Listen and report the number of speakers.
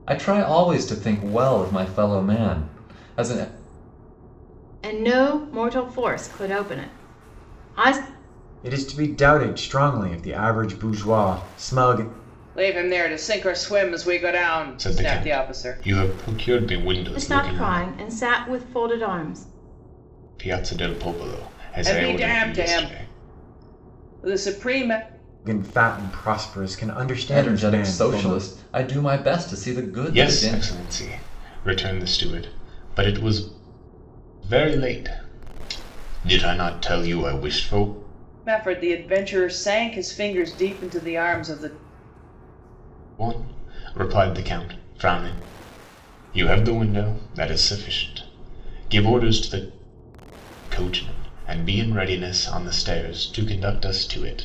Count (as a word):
five